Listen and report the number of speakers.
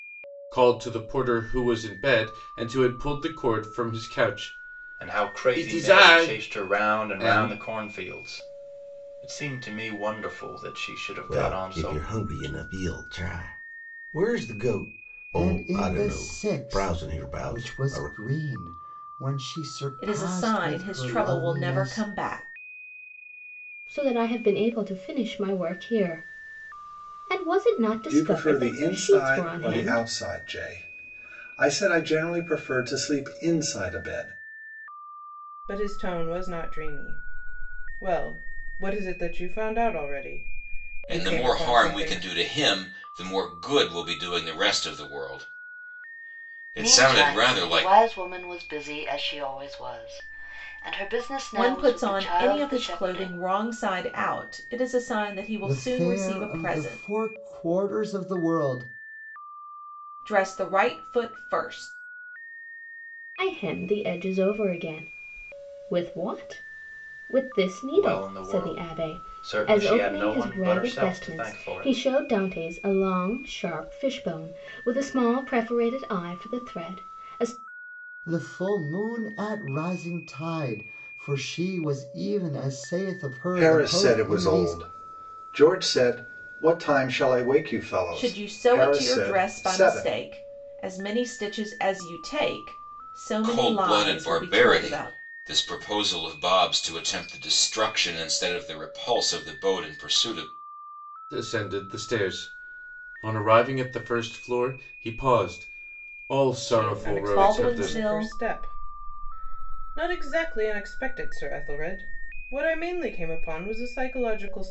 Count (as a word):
ten